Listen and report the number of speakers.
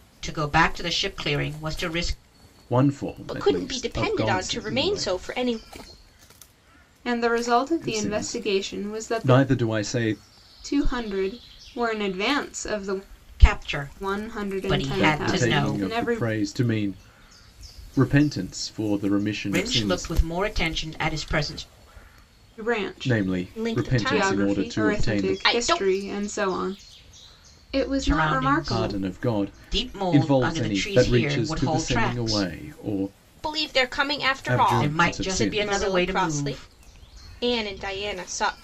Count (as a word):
four